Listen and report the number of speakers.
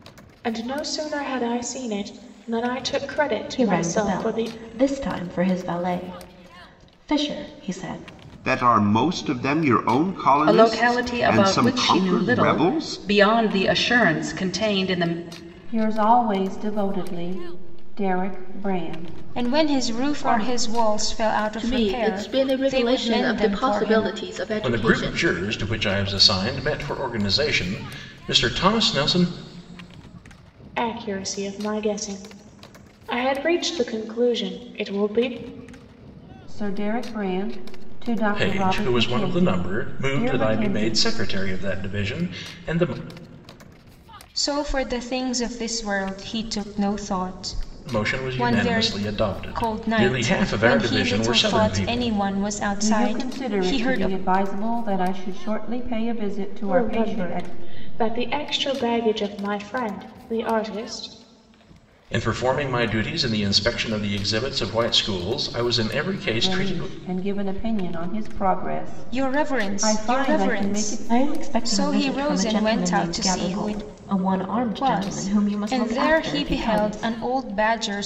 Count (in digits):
8